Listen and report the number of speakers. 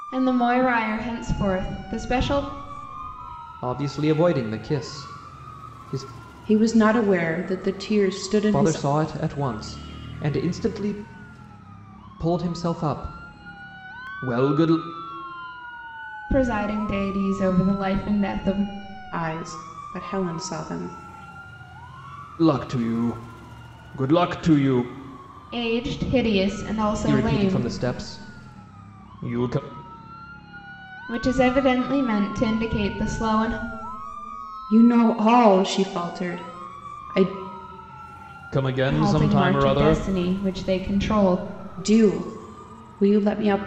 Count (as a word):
three